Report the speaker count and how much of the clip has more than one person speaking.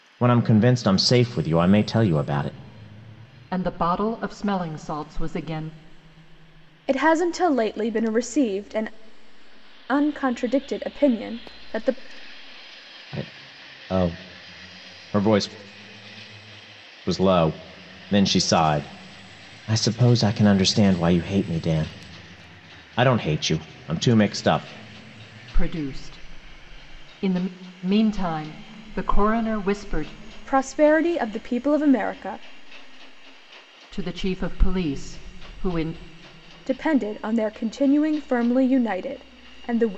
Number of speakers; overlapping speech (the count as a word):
three, no overlap